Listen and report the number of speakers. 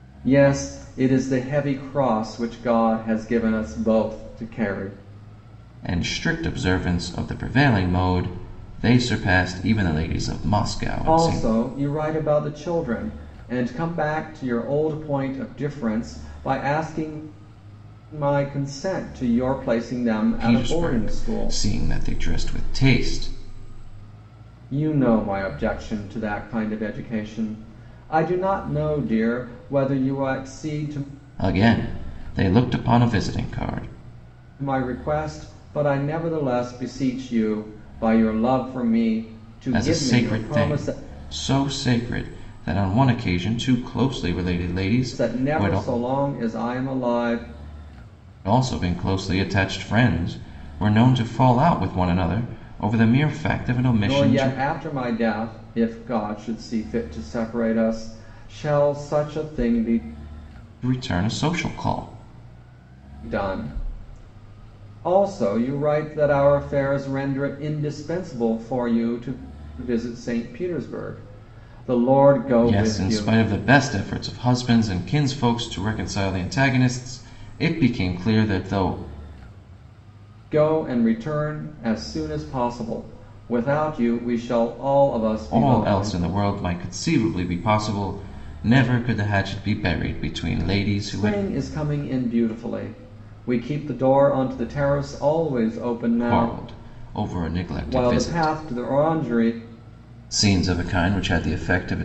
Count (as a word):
two